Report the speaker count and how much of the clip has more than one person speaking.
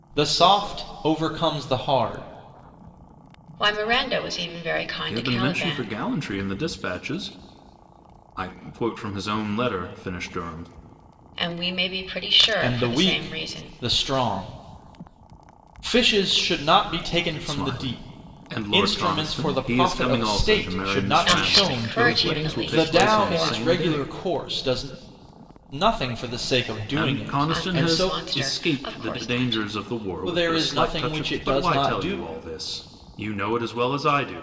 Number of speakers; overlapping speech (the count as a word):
three, about 37%